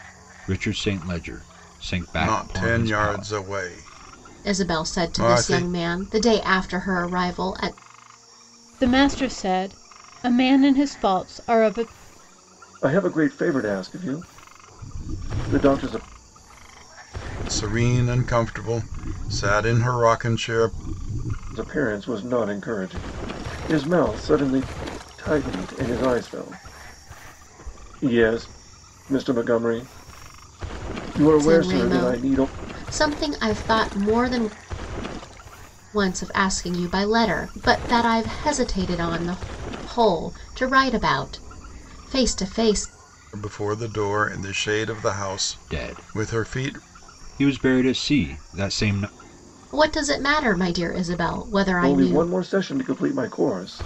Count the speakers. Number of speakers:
five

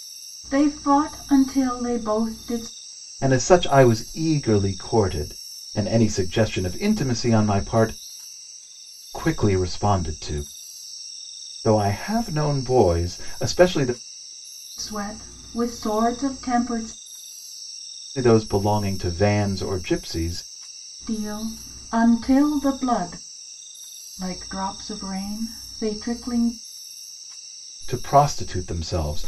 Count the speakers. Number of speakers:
two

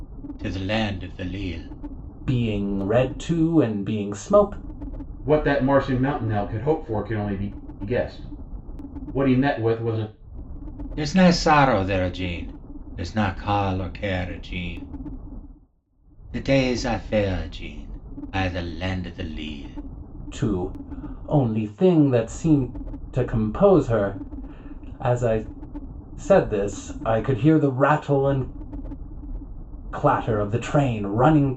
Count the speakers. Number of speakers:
three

